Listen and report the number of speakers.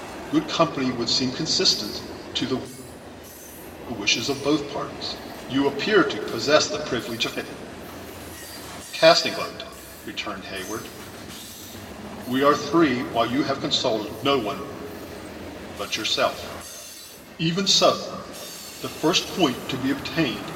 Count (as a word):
one